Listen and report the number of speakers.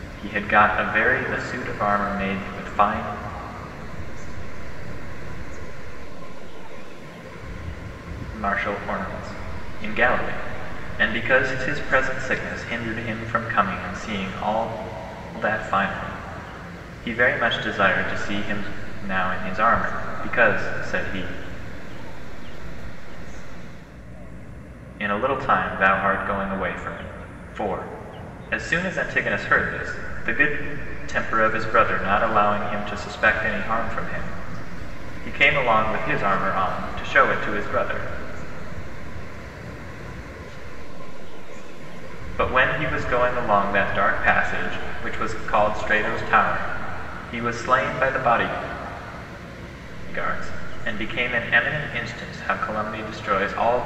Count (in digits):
2